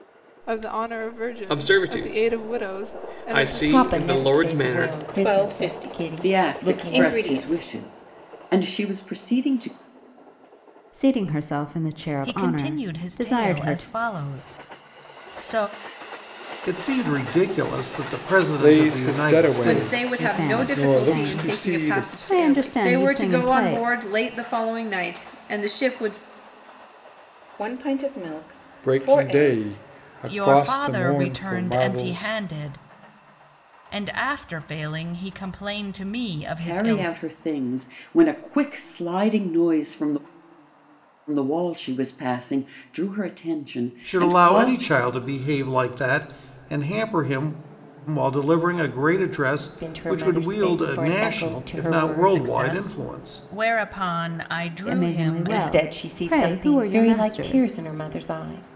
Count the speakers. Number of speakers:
10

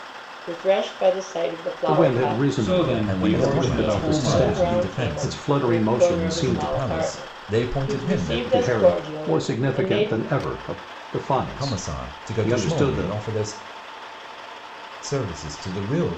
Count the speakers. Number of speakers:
4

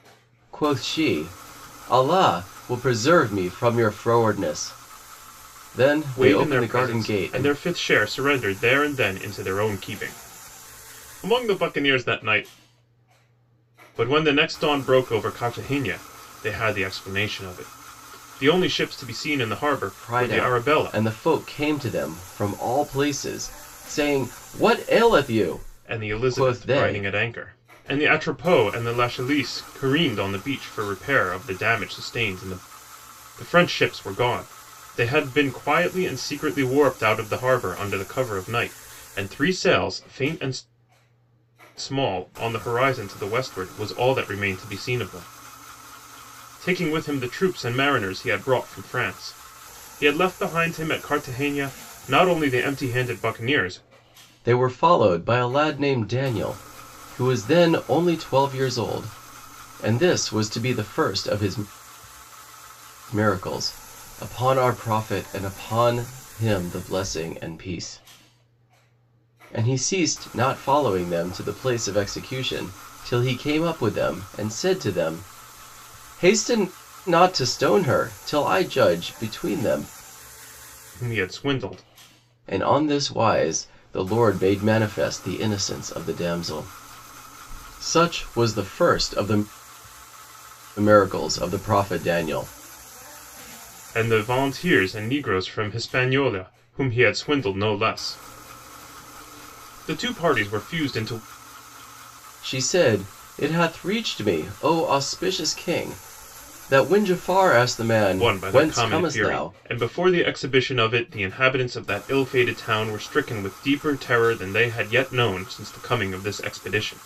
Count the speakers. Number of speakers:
2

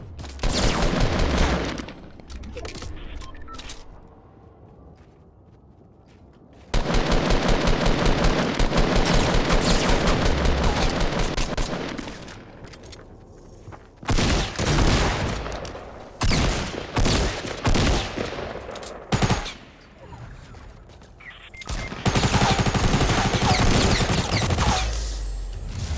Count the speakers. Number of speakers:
0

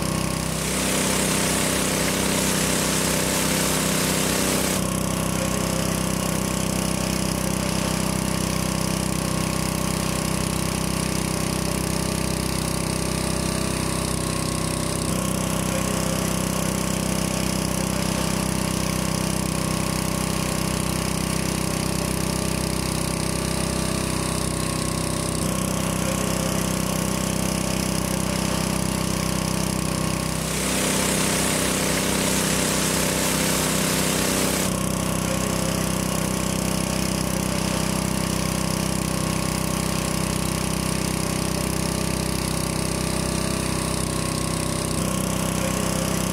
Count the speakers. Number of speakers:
0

